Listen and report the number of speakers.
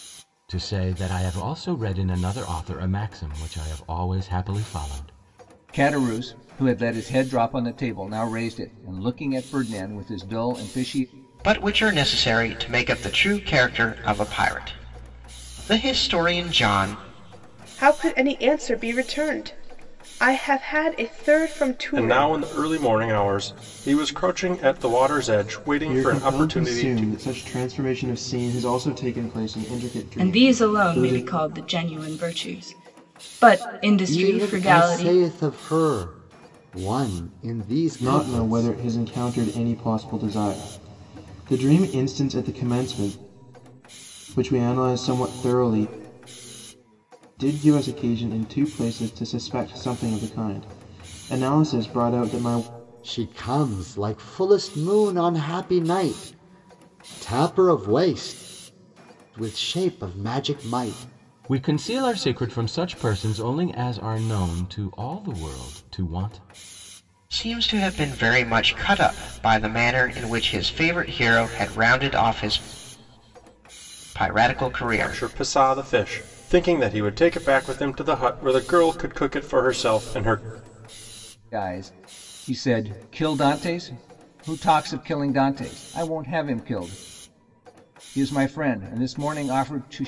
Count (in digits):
8